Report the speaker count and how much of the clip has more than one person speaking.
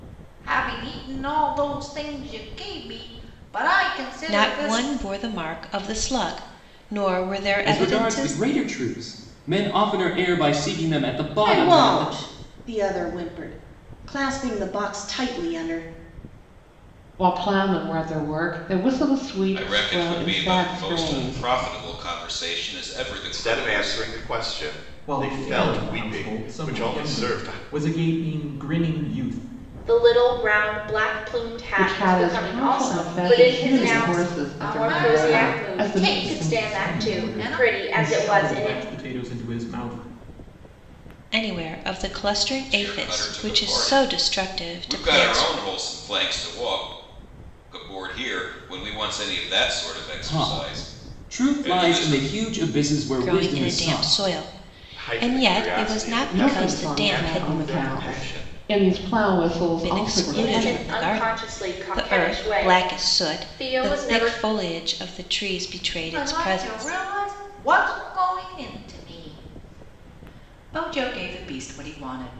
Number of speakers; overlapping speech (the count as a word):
nine, about 41%